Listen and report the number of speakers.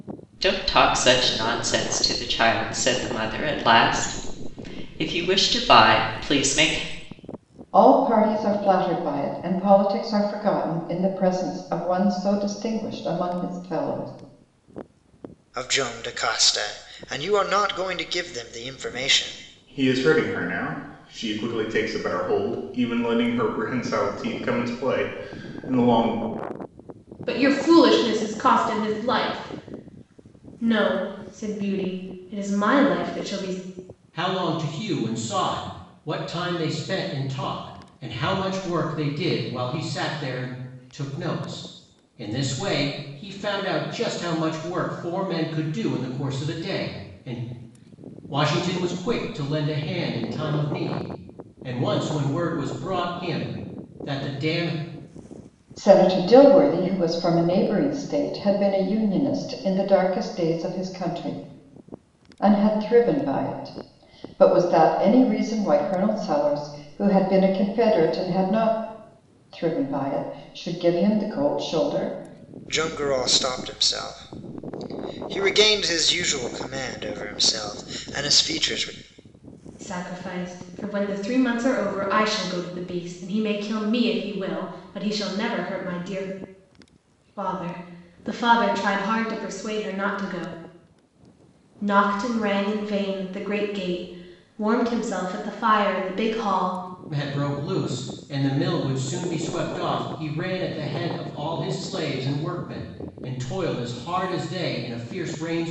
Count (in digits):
6